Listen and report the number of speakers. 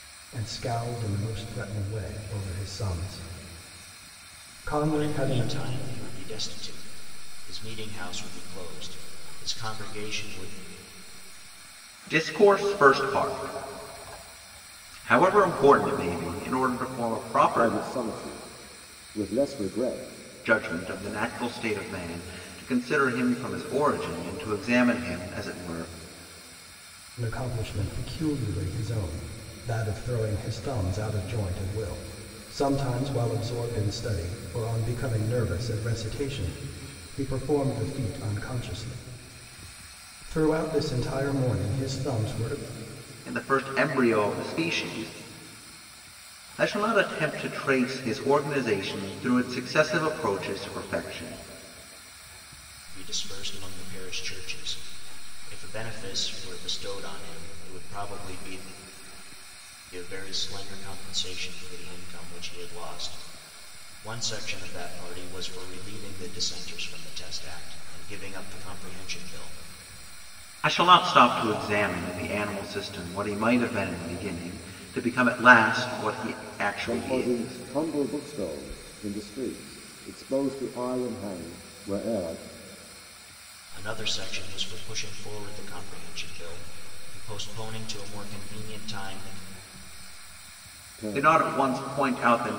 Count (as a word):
four